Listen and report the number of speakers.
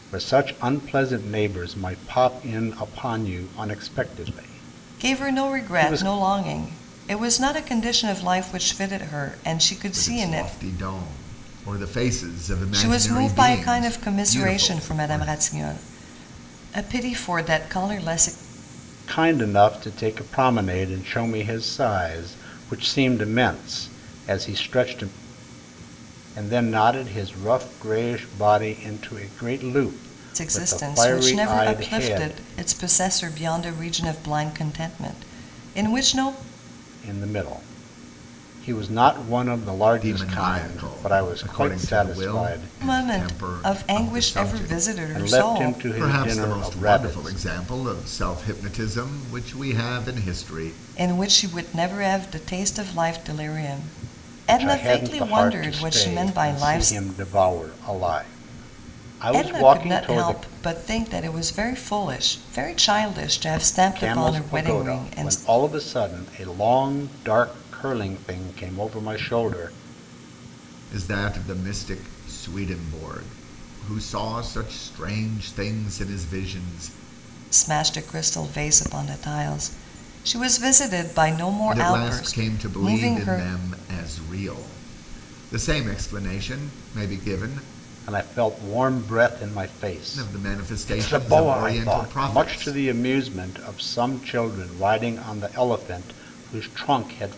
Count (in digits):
3